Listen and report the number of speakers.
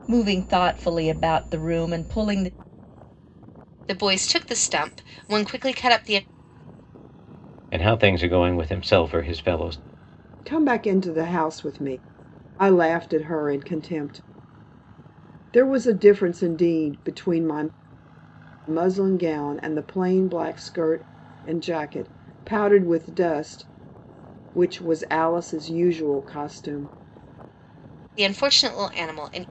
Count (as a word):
four